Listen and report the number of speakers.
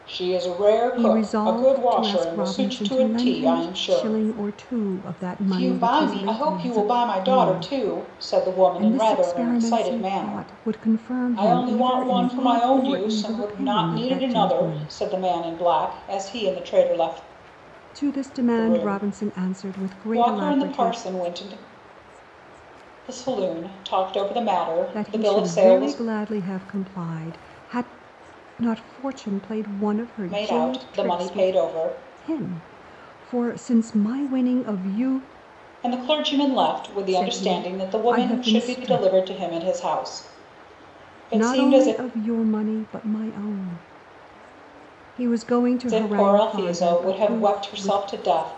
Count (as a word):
two